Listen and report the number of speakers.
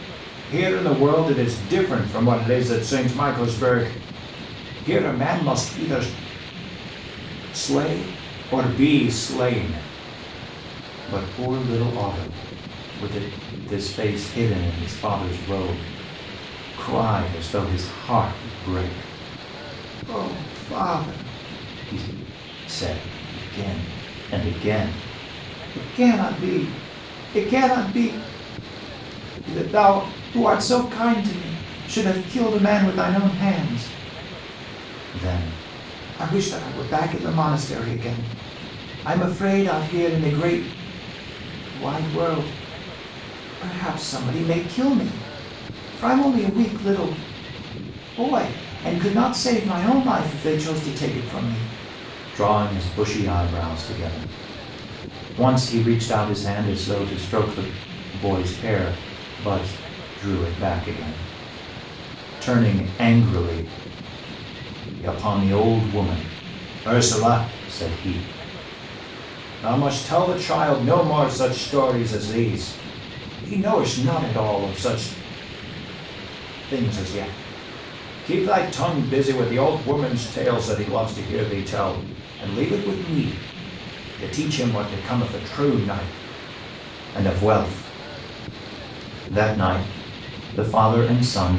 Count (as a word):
one